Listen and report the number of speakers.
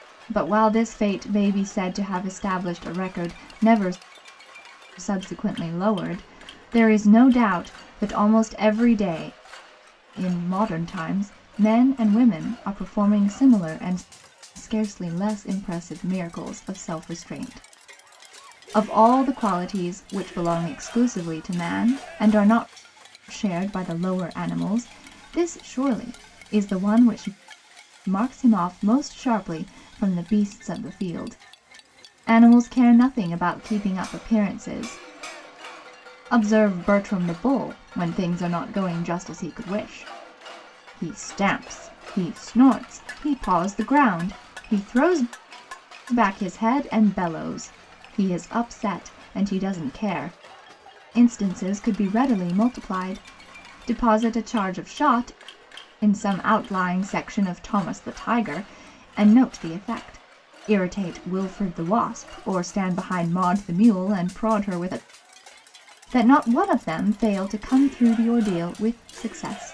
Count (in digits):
1